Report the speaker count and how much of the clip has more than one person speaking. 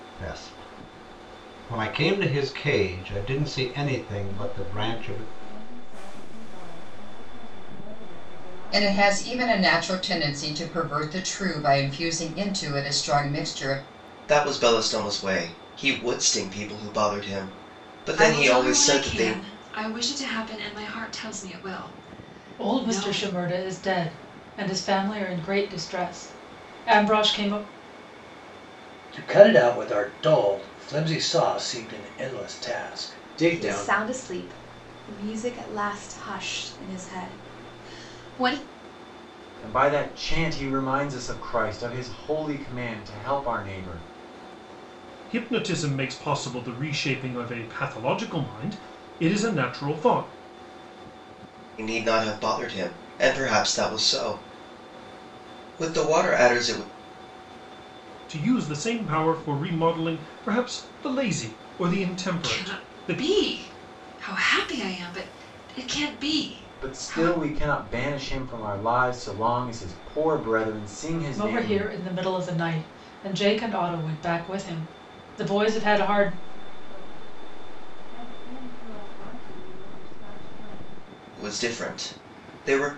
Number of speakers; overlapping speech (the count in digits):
10, about 8%